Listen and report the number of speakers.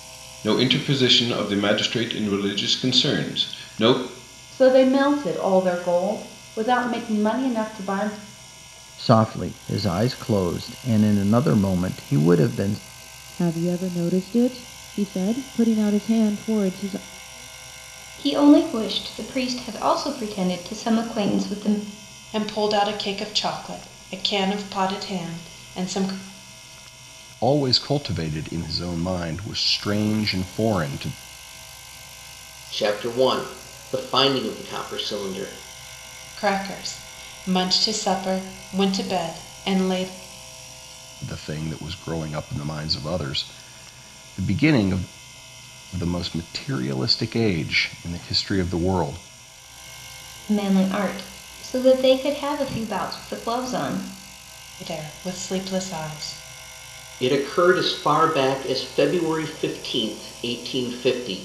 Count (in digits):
8